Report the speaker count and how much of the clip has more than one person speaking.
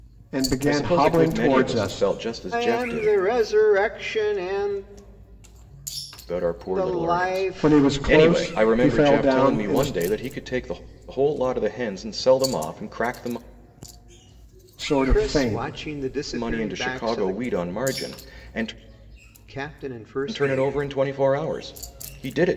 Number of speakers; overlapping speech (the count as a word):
three, about 34%